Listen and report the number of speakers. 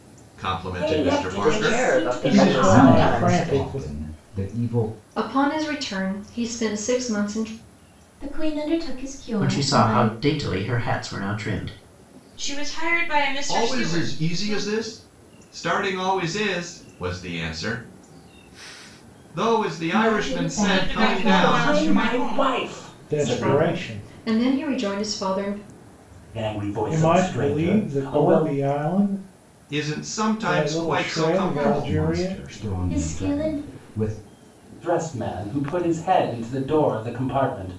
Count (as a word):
nine